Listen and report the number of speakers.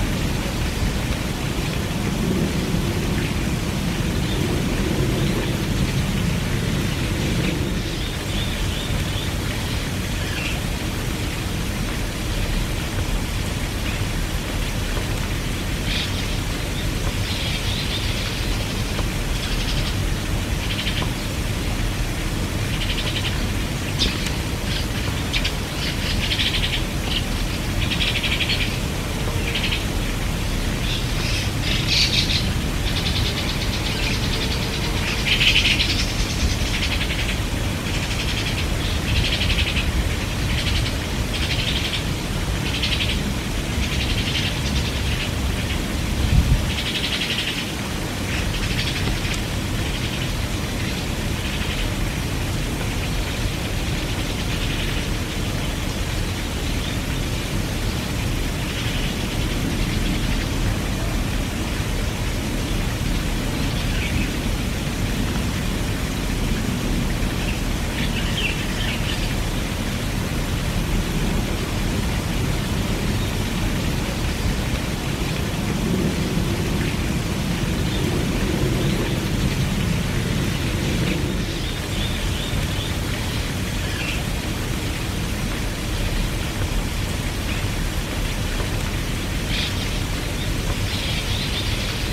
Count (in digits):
0